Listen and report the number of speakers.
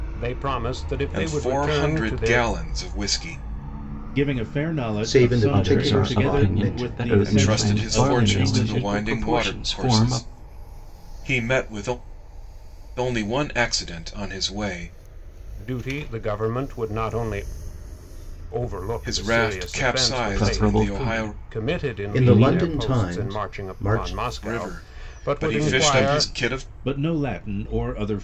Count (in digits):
5